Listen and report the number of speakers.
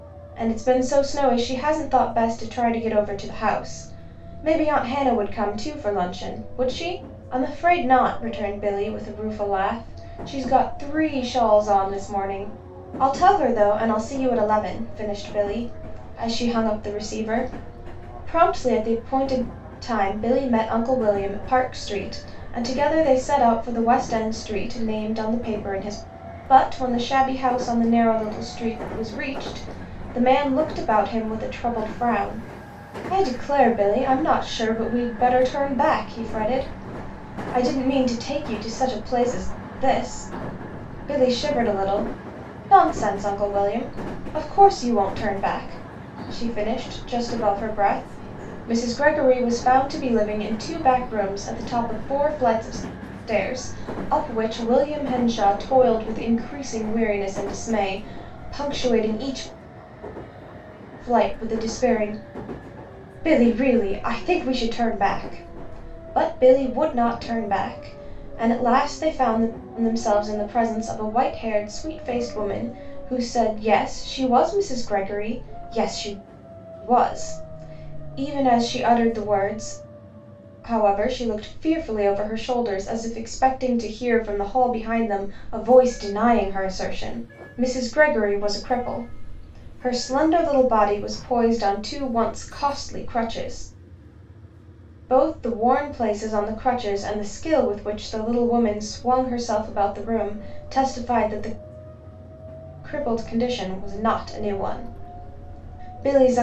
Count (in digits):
1